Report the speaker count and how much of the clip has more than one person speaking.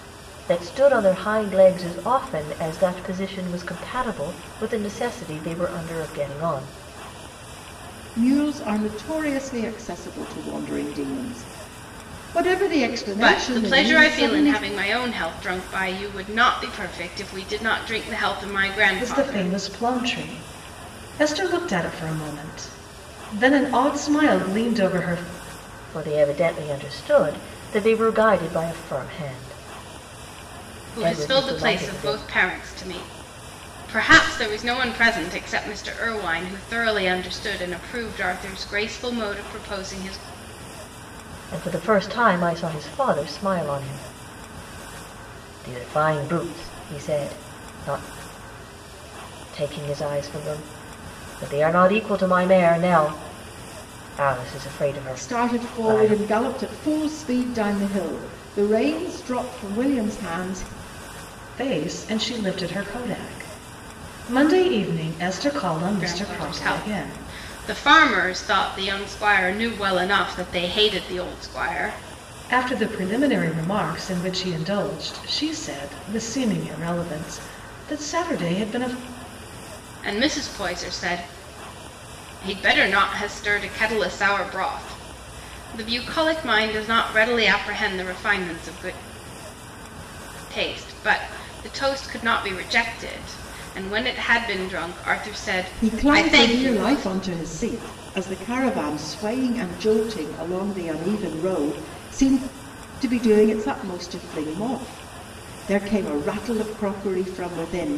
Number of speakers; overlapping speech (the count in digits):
4, about 7%